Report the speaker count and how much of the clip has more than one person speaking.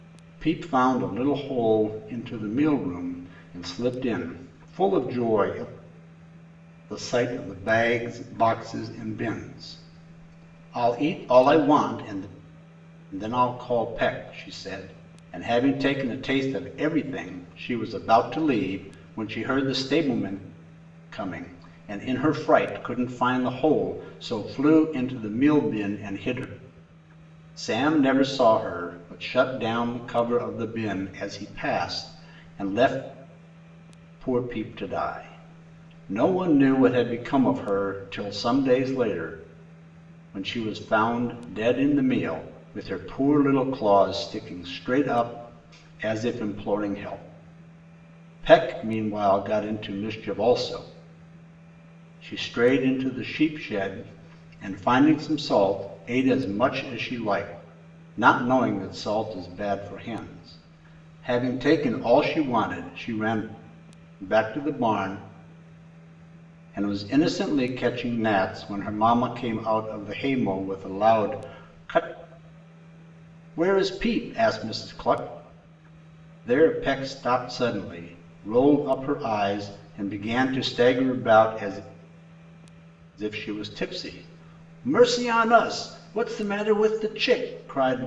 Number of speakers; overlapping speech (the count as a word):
one, no overlap